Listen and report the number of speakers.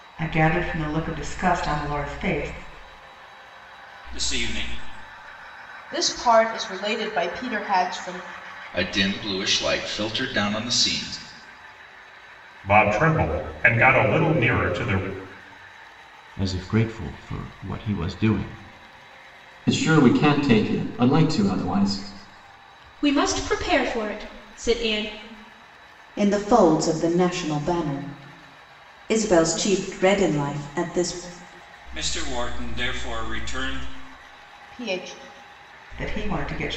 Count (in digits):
9